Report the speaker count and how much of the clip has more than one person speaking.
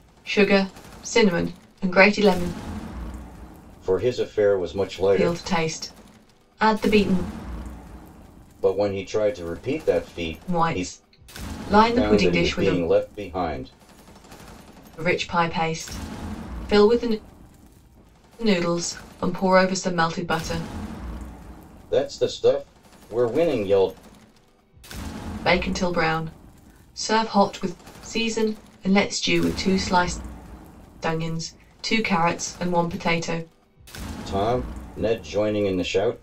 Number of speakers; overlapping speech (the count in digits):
2, about 5%